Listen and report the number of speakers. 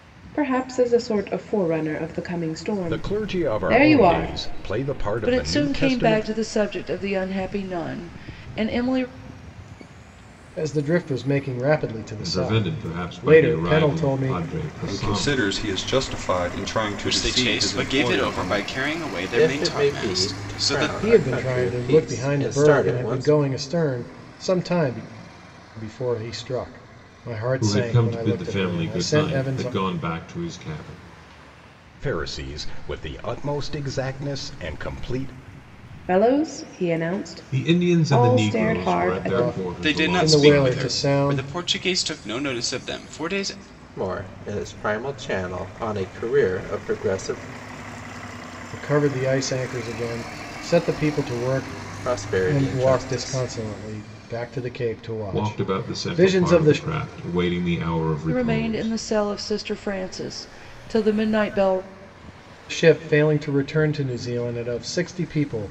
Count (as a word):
eight